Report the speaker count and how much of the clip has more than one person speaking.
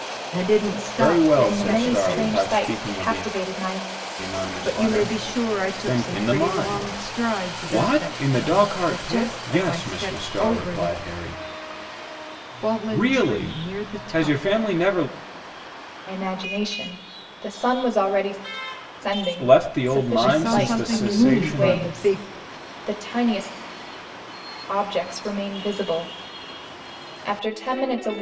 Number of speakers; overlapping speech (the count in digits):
3, about 47%